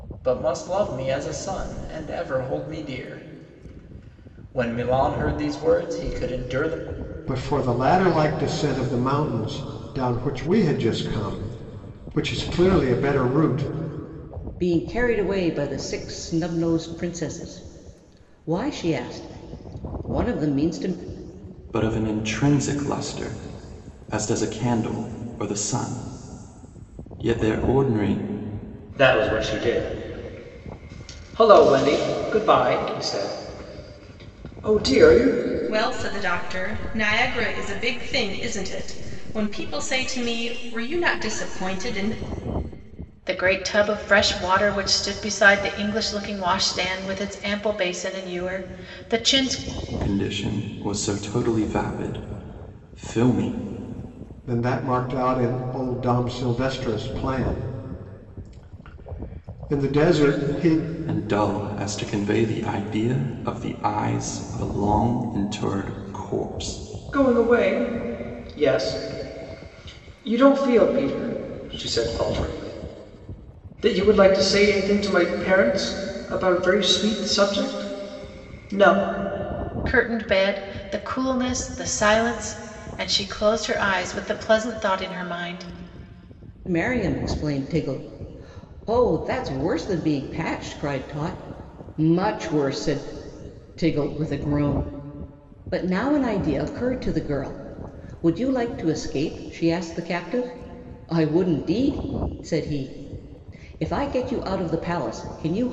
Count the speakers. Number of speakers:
7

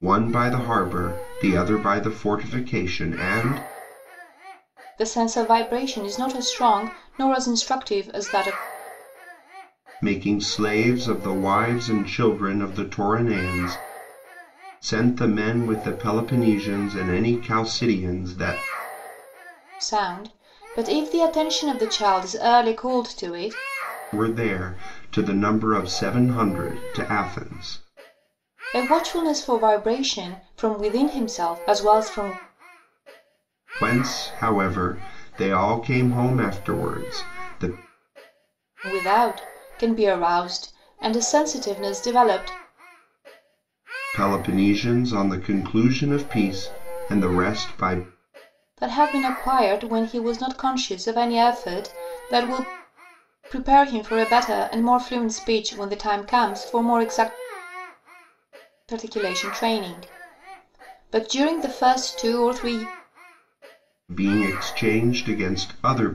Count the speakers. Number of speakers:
2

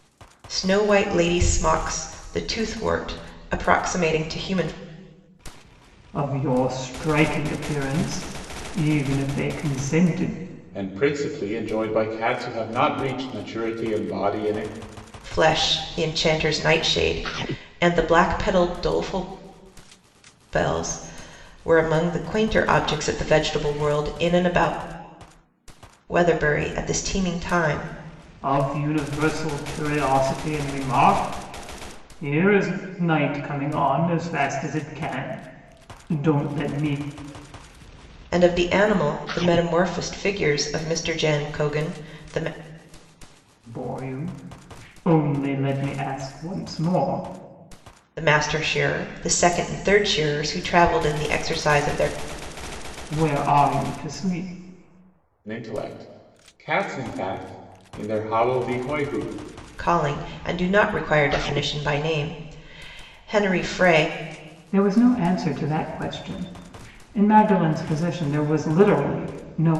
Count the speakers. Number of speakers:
3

